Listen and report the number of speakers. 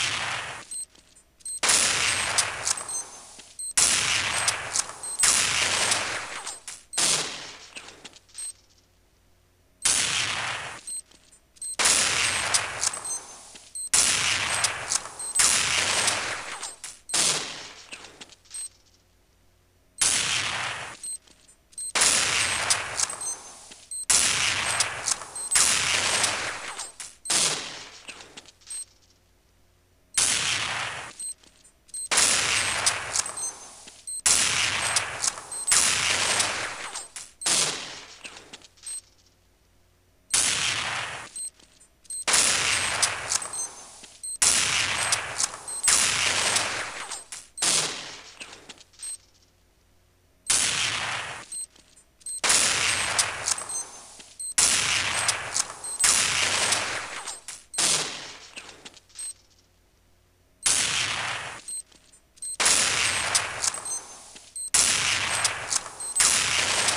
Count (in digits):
0